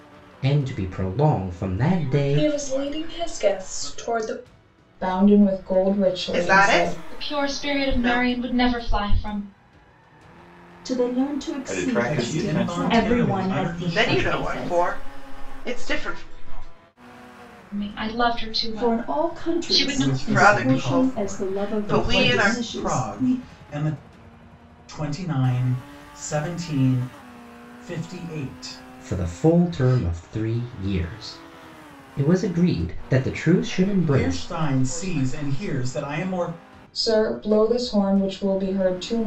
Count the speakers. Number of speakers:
ten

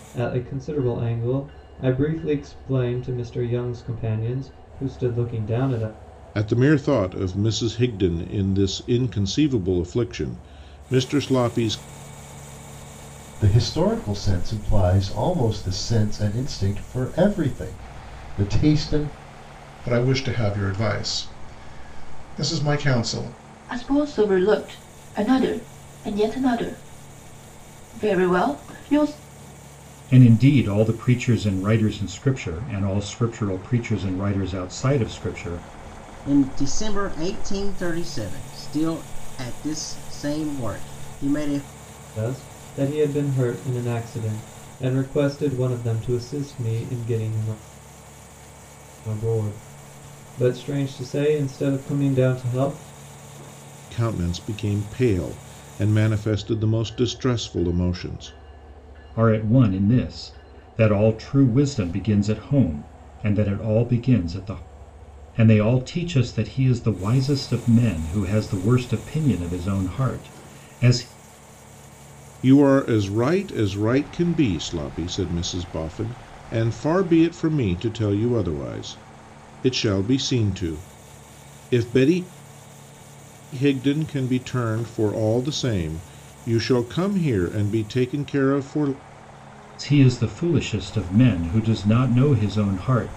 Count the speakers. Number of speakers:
seven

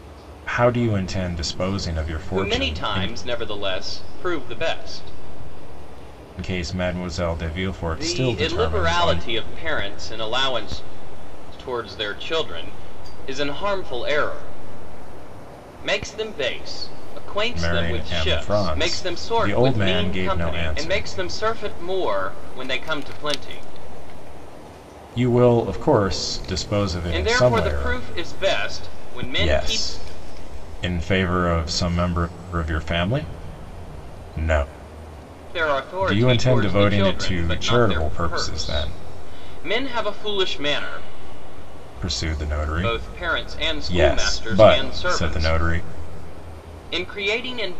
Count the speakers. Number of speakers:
two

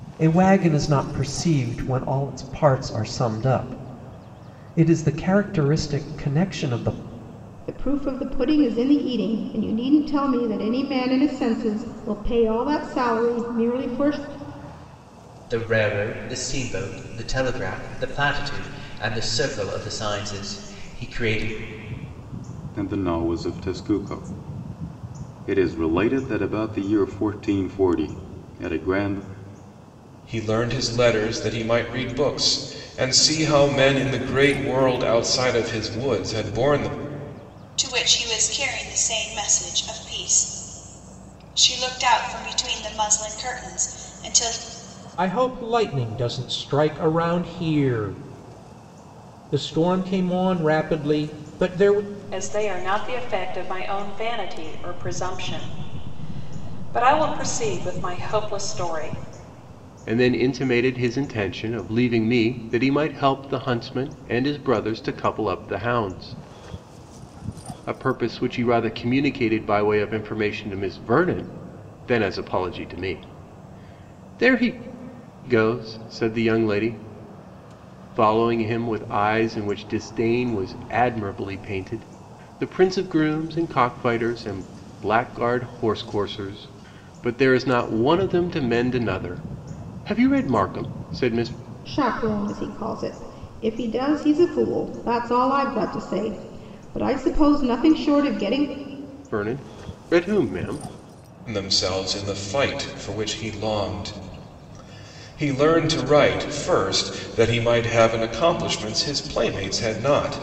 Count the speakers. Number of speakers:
nine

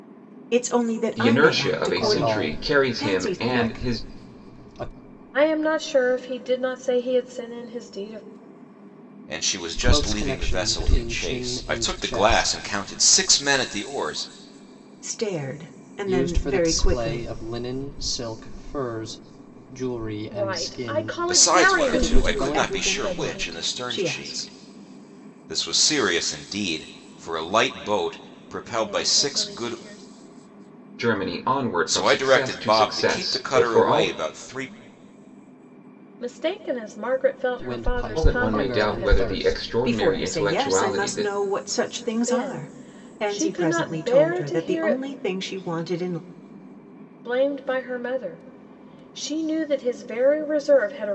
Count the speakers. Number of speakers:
five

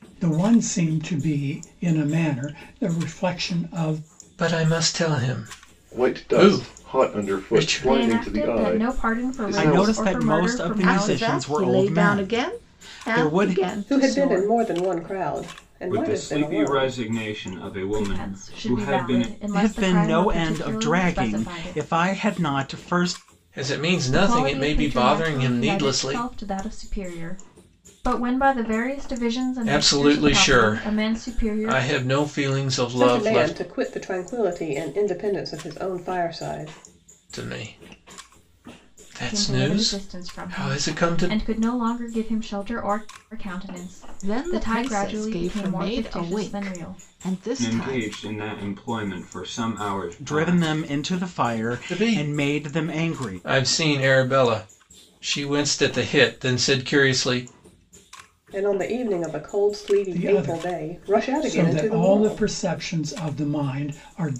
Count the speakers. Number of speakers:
eight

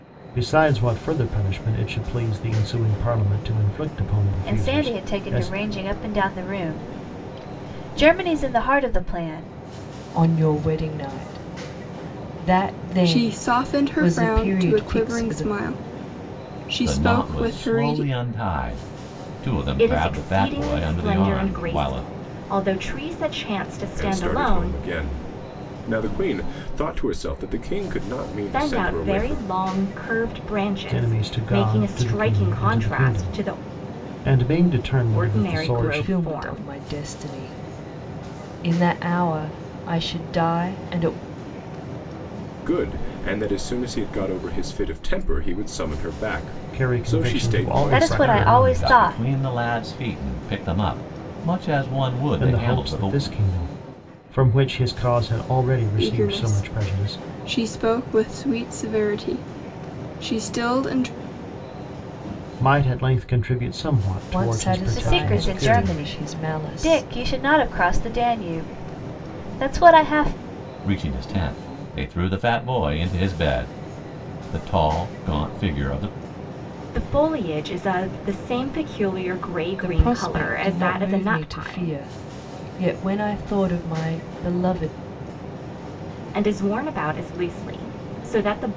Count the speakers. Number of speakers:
seven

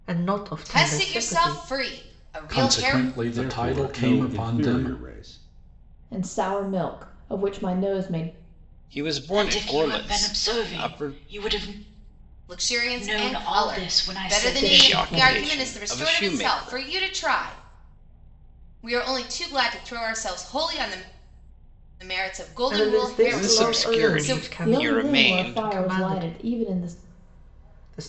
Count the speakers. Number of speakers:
seven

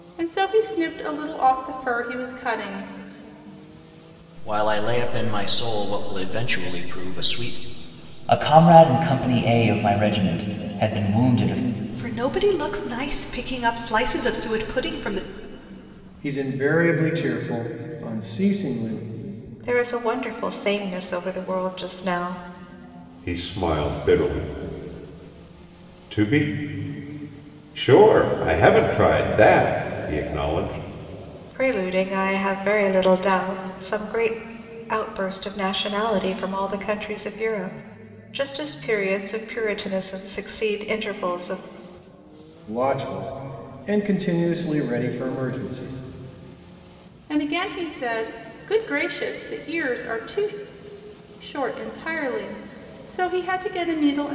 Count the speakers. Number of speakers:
seven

